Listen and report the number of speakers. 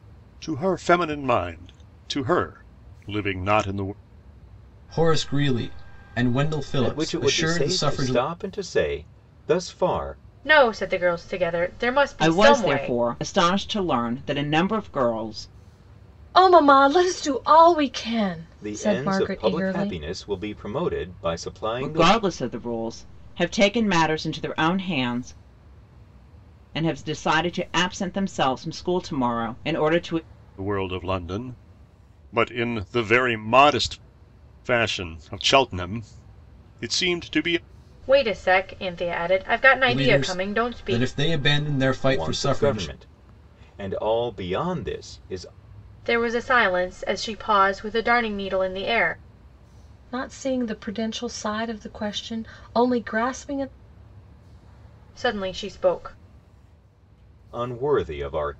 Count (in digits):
6